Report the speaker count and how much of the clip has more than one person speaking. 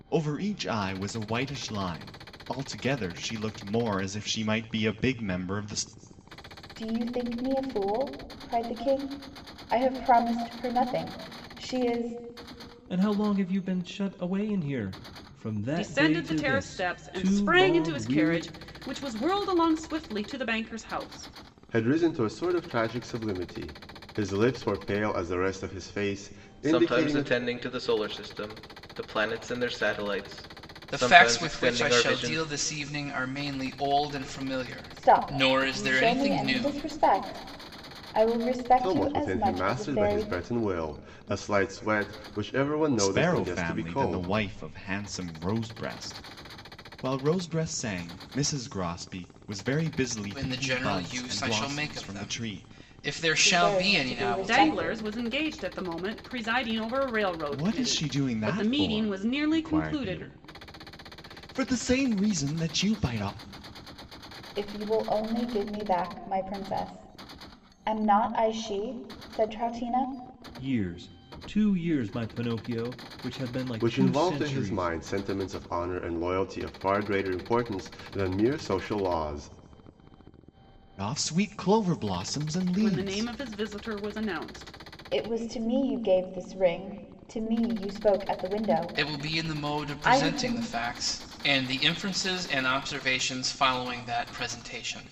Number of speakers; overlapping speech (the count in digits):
7, about 21%